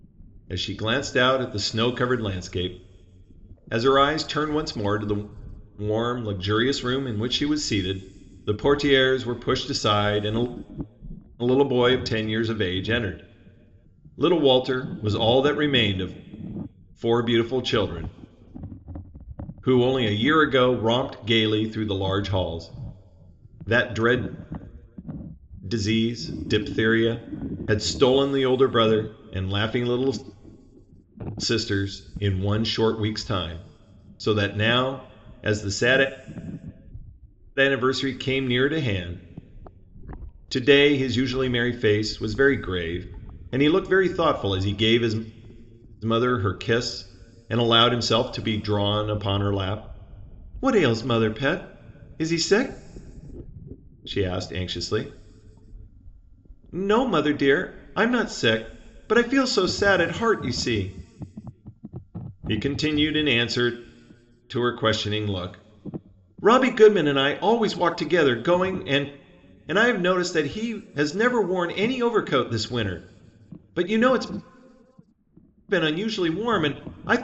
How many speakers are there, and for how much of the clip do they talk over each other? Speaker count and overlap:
one, no overlap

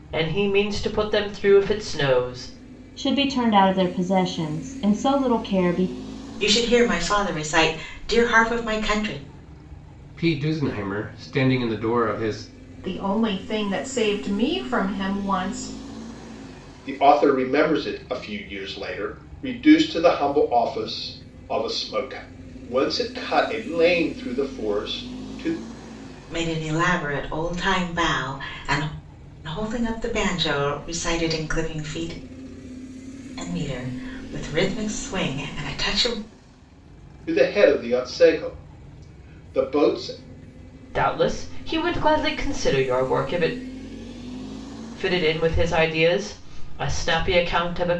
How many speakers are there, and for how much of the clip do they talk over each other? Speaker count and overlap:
six, no overlap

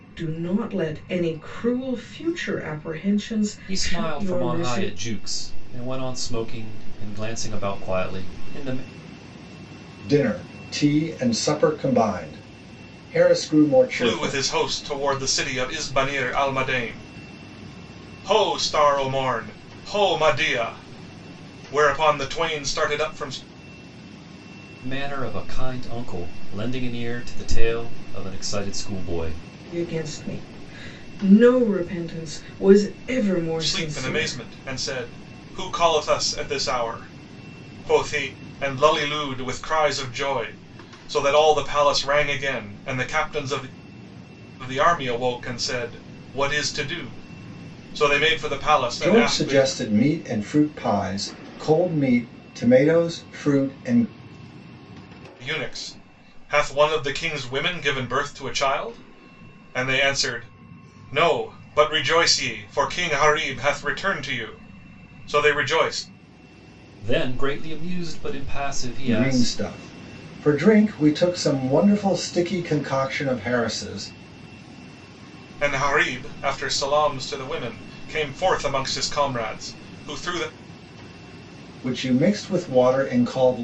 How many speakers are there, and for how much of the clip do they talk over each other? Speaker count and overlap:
four, about 5%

